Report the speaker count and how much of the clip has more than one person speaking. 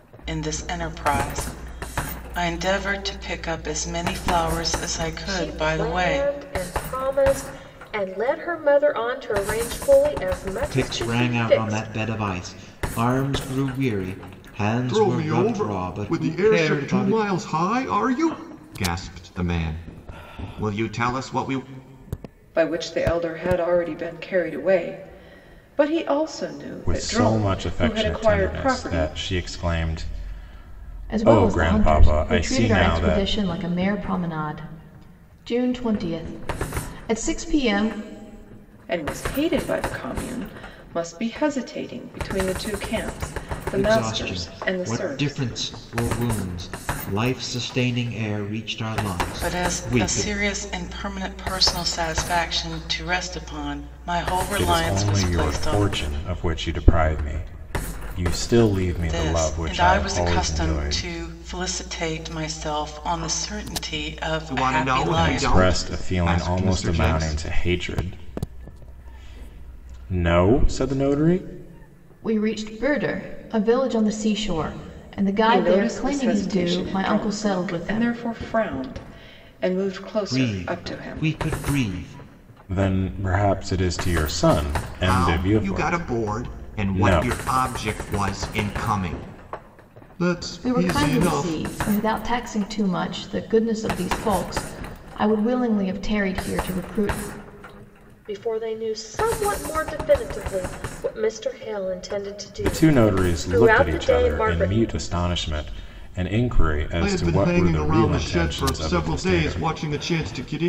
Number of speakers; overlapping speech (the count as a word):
seven, about 27%